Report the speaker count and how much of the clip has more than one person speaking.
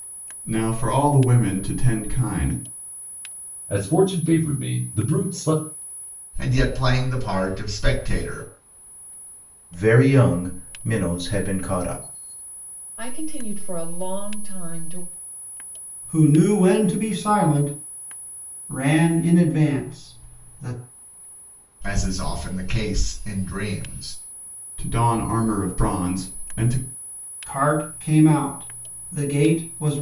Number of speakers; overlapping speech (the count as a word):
six, no overlap